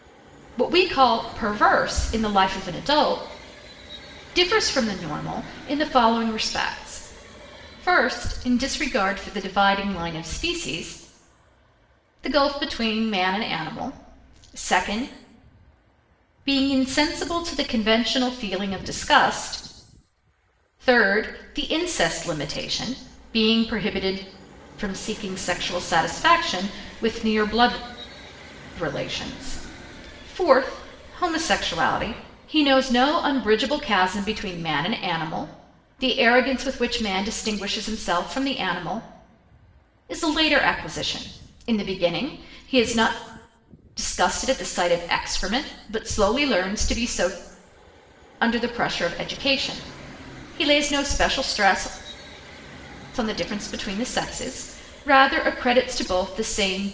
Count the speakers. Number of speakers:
1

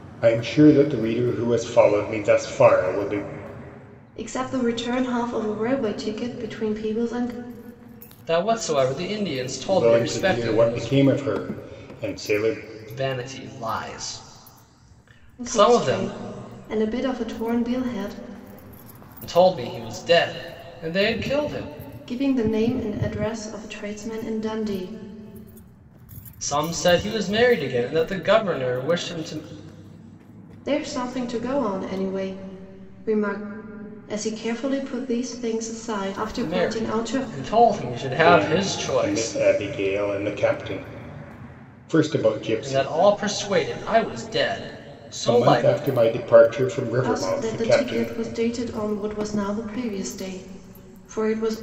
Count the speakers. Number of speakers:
3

